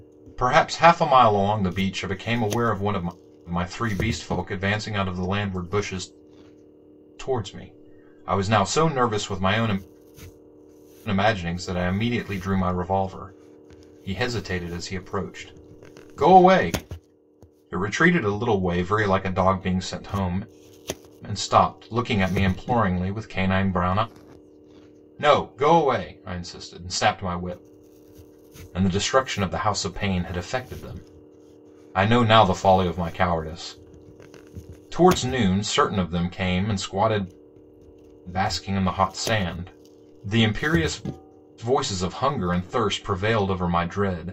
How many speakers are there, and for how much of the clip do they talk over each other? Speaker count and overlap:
1, no overlap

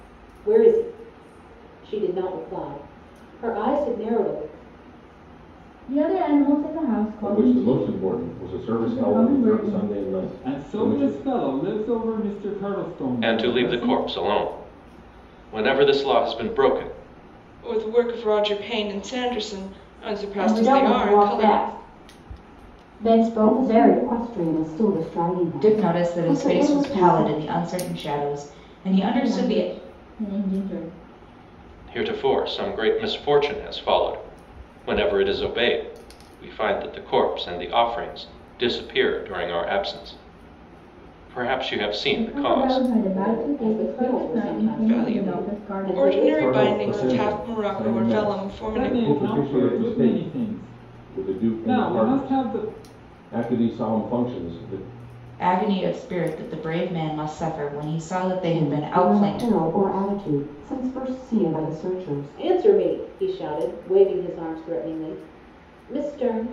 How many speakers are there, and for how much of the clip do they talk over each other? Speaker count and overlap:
9, about 31%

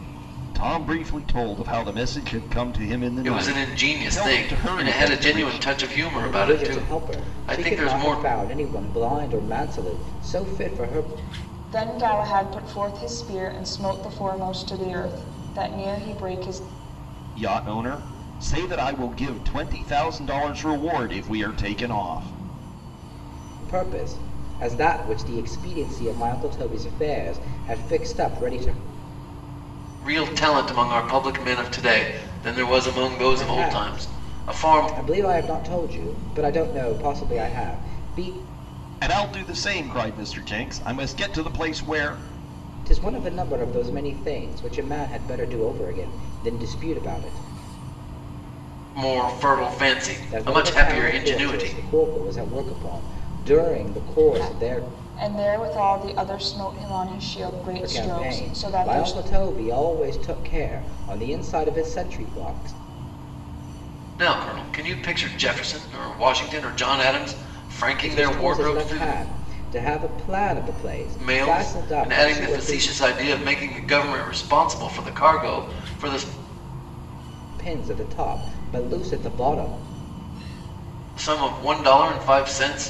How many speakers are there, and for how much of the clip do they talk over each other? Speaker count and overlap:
4, about 15%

